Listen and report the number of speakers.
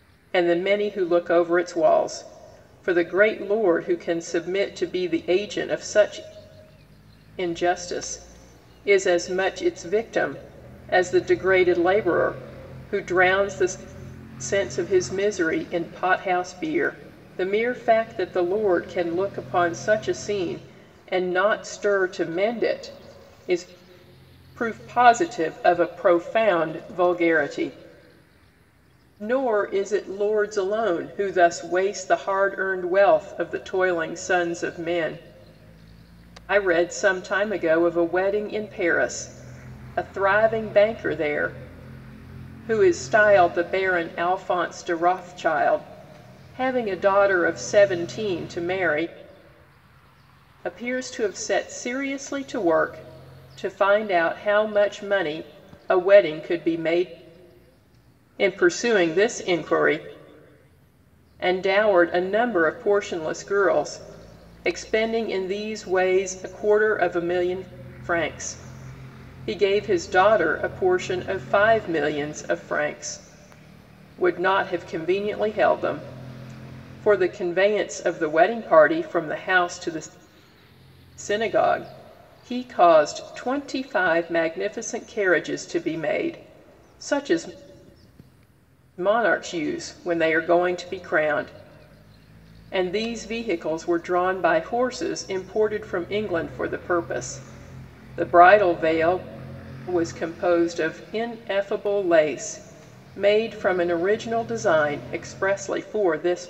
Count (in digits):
1